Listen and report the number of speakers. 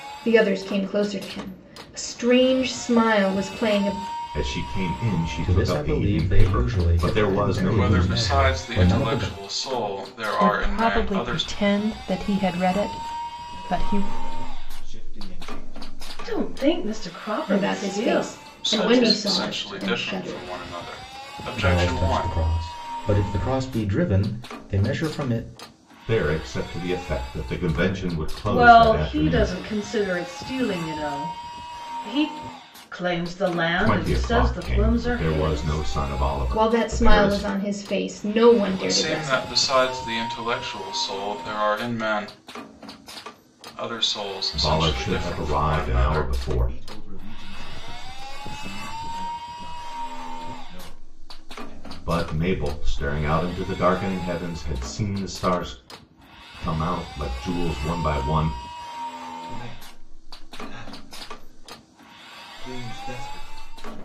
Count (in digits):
7